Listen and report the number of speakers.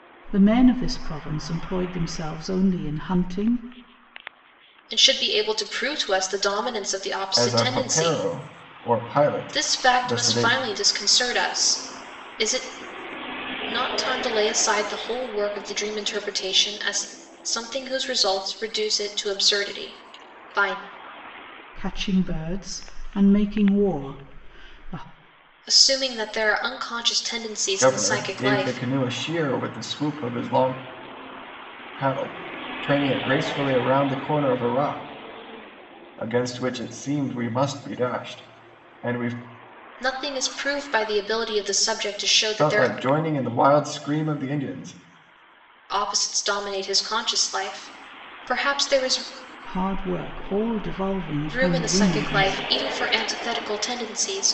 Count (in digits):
3